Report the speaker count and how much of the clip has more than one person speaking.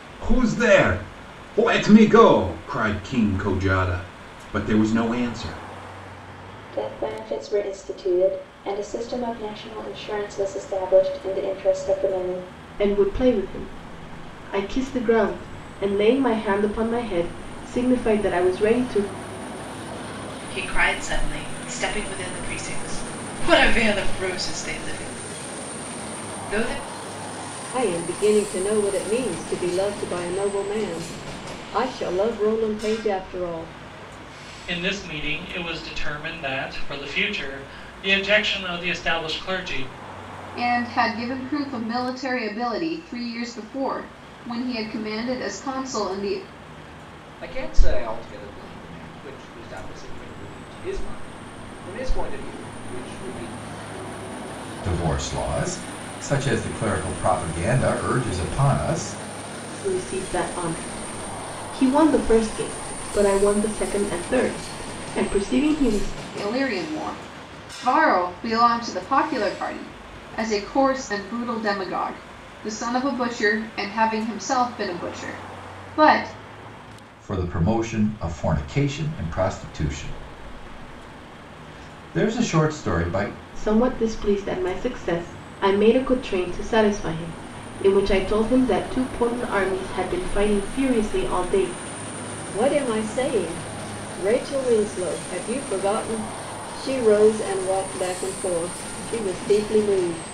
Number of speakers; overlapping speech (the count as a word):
nine, no overlap